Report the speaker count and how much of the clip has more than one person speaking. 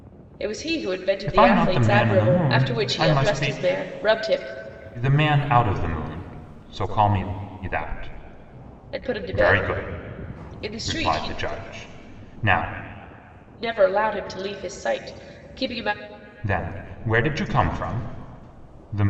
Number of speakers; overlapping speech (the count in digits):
2, about 21%